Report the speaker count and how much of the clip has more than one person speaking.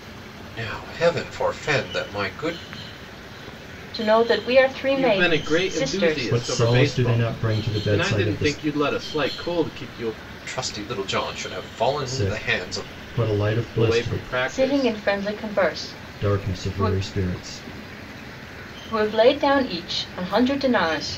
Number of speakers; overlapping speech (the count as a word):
four, about 27%